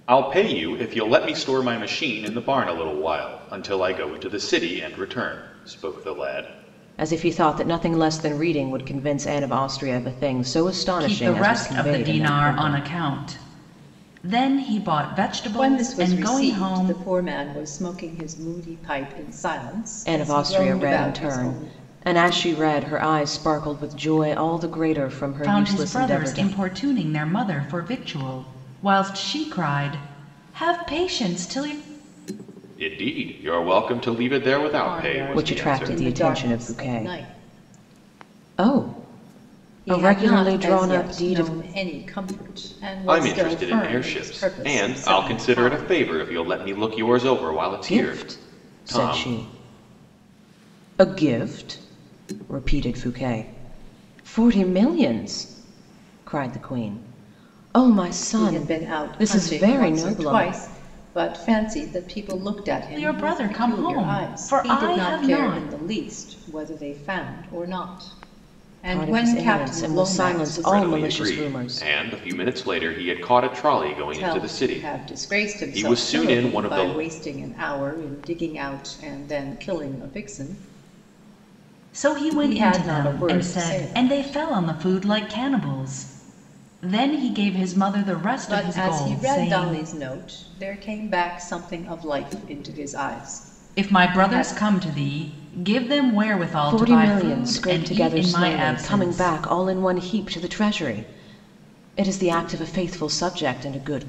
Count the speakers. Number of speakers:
4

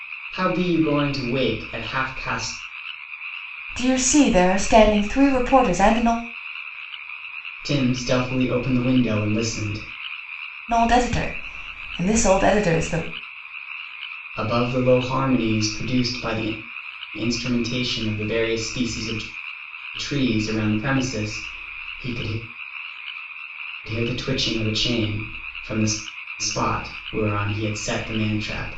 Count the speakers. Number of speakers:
2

